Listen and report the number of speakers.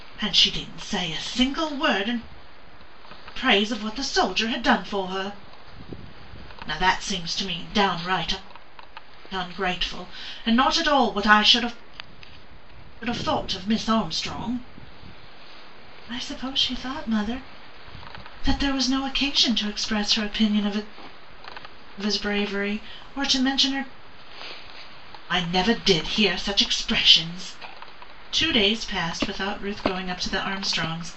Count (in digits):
1